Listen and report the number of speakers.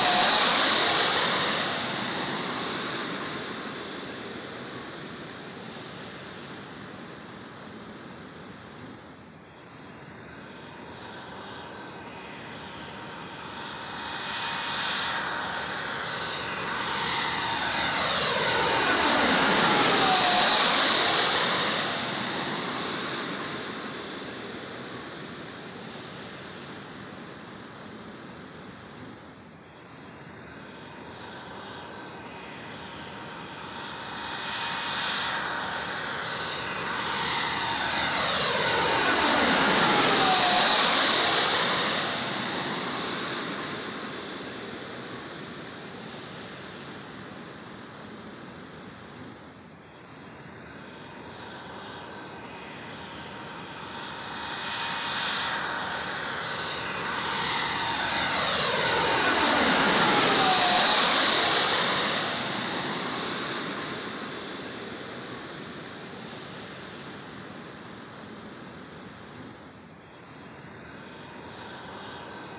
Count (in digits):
0